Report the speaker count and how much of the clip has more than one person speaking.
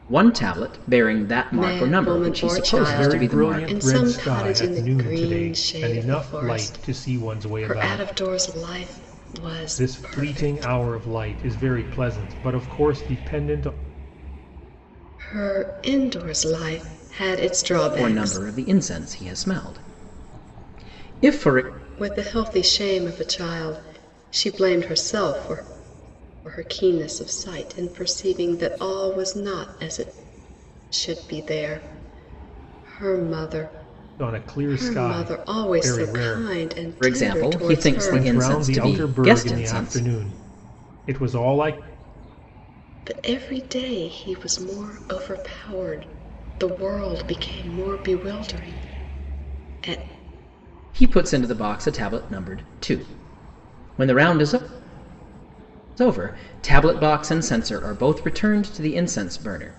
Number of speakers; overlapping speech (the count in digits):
3, about 24%